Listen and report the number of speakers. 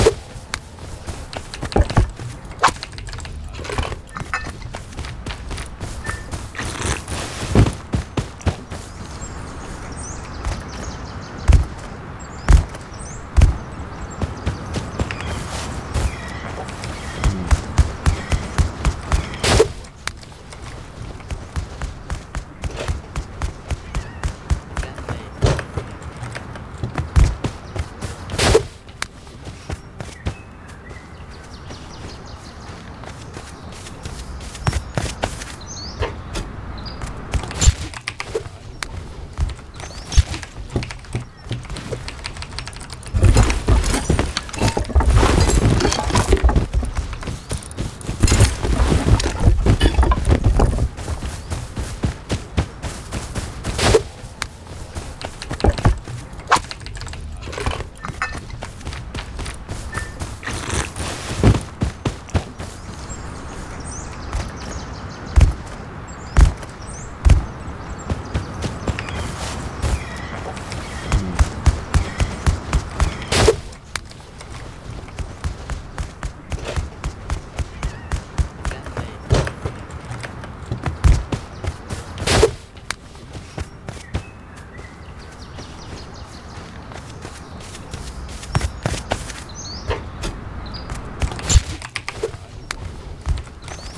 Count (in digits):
0